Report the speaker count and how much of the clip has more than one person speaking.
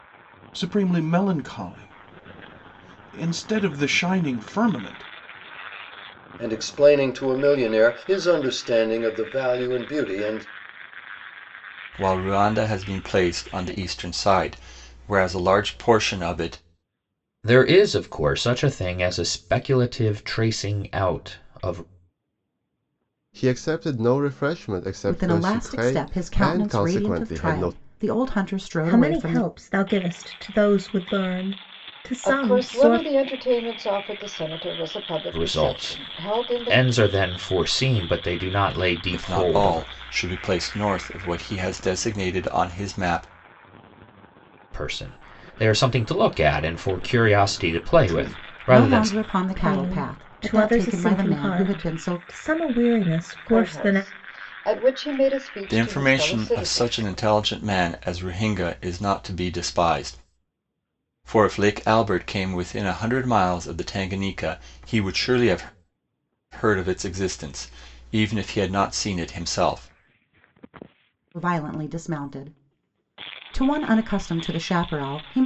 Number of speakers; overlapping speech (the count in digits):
8, about 17%